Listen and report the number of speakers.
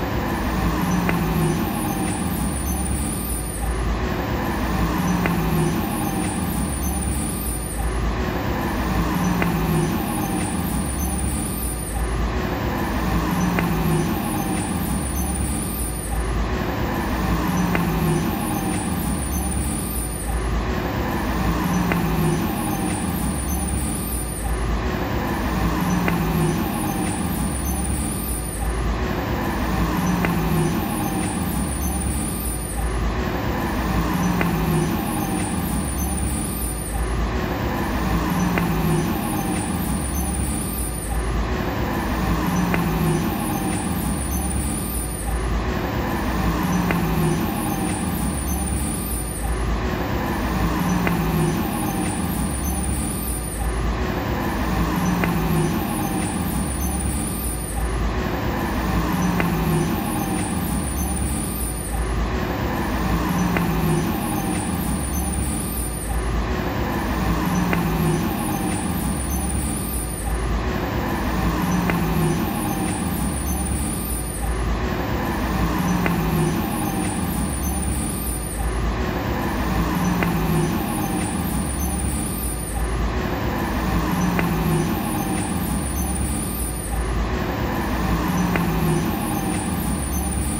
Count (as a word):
zero